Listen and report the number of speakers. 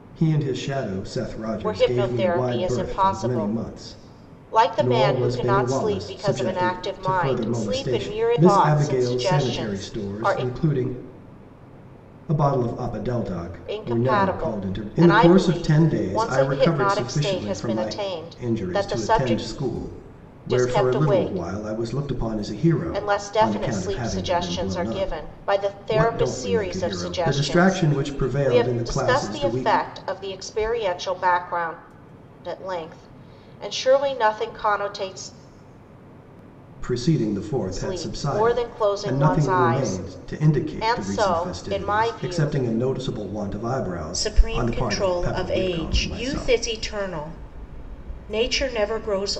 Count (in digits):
2